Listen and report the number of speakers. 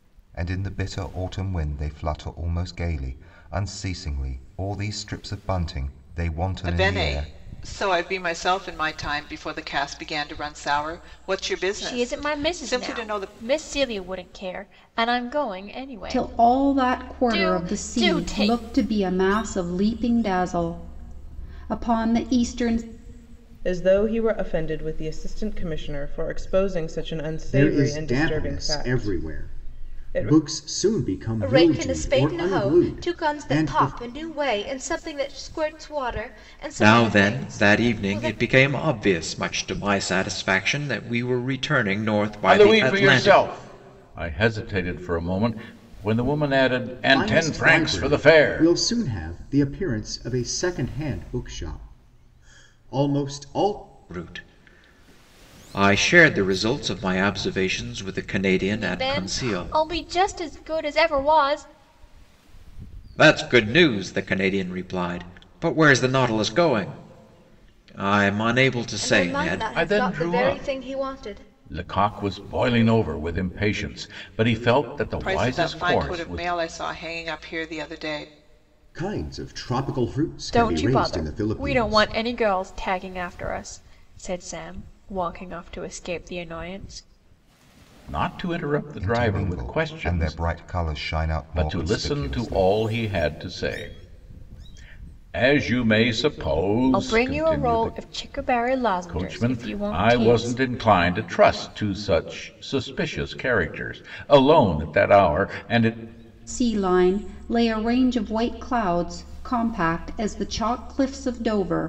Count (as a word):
nine